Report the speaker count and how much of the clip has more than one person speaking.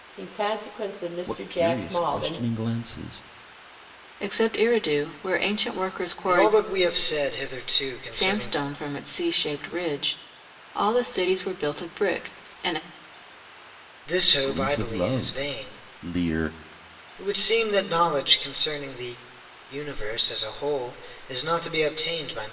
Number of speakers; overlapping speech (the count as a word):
four, about 16%